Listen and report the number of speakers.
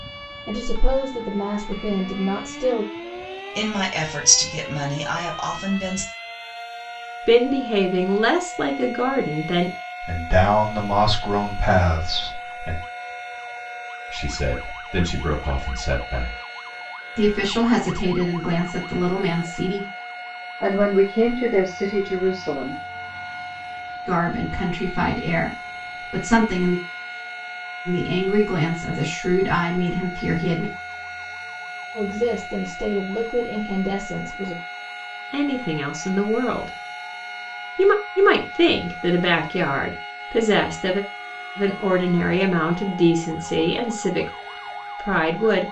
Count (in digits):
7